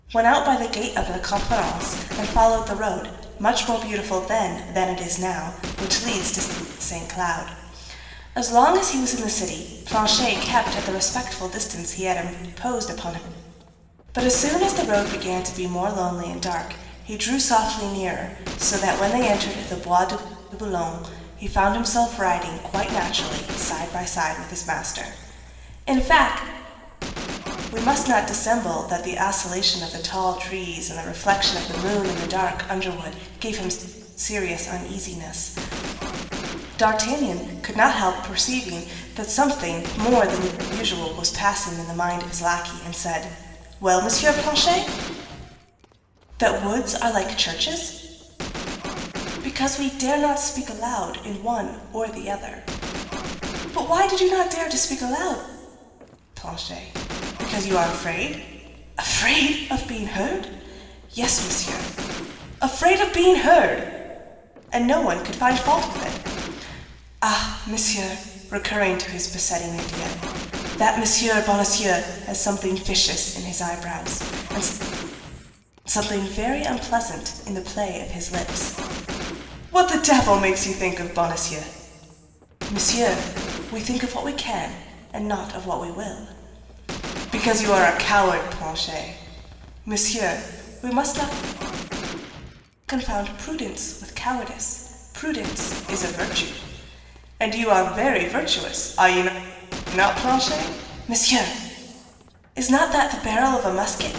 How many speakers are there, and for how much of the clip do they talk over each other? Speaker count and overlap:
1, no overlap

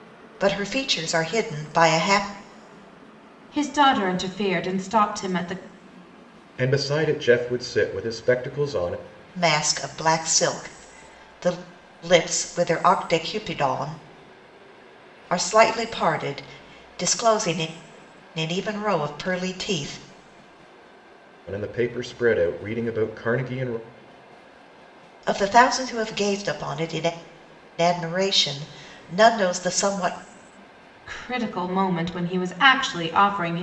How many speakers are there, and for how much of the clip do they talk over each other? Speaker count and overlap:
3, no overlap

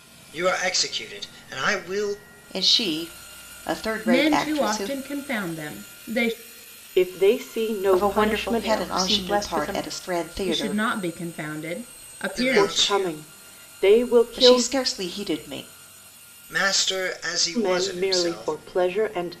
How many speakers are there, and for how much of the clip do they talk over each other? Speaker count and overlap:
5, about 29%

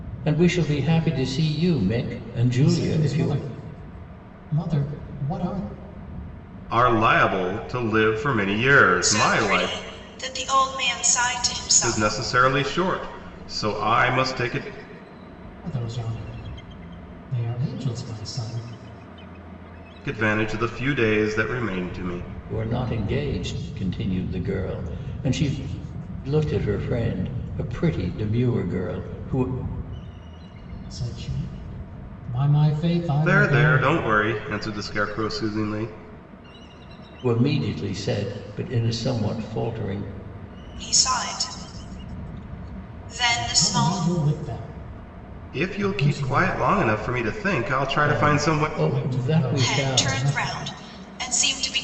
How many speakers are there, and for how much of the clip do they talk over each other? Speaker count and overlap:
4, about 14%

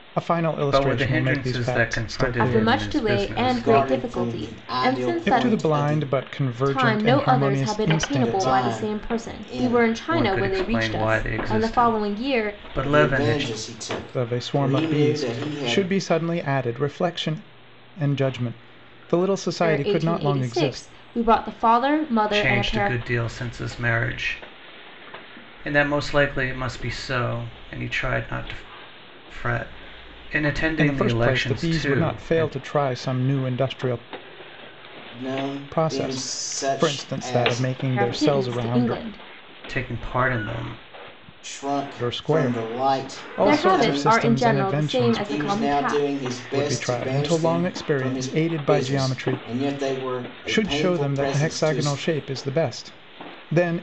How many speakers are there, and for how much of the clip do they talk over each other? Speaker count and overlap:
4, about 53%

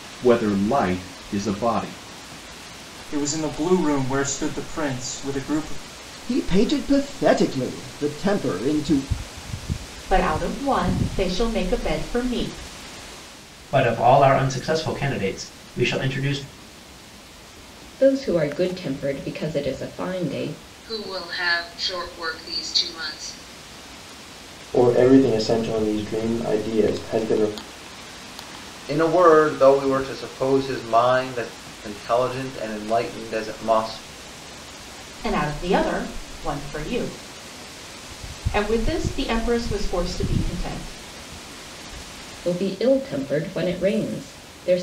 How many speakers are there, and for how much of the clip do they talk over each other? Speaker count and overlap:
9, no overlap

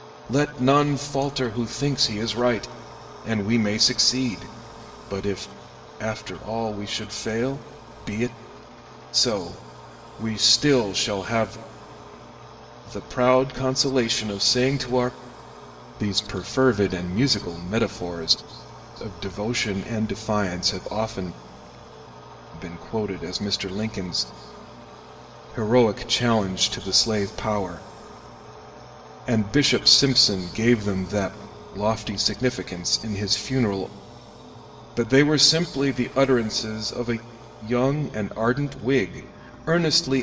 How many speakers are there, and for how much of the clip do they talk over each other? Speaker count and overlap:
1, no overlap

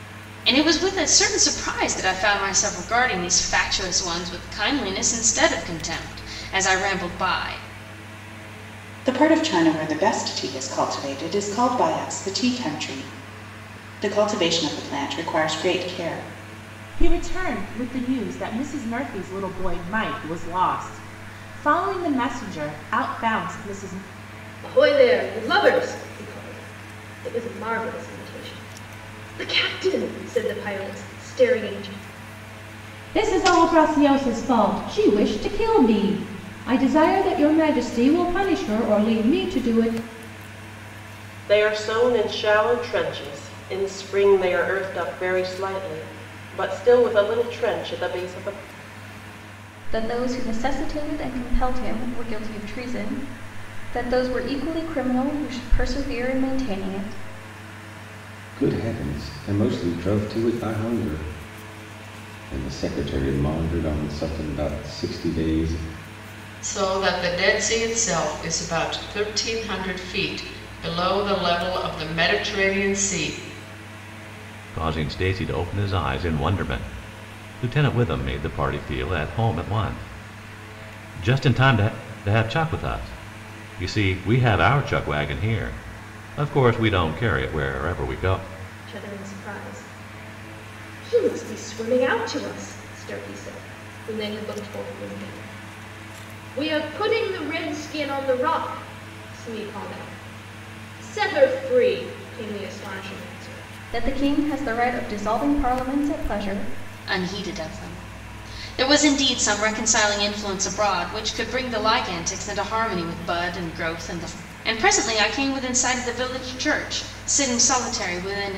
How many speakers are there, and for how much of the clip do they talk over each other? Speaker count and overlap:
10, no overlap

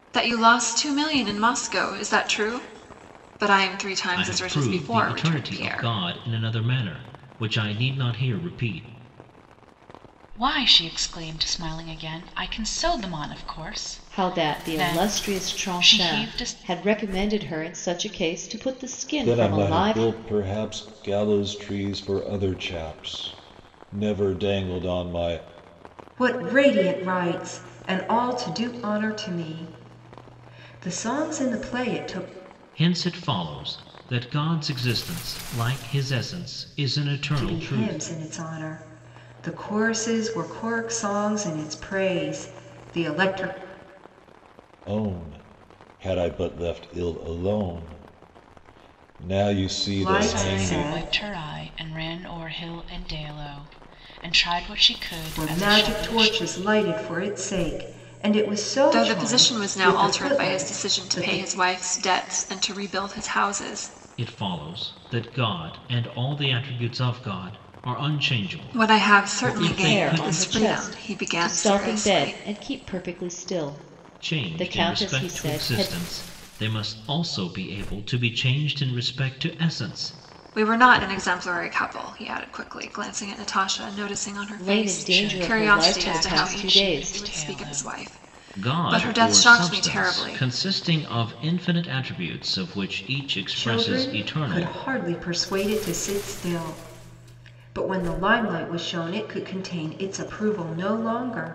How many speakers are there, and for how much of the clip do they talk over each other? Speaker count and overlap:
6, about 22%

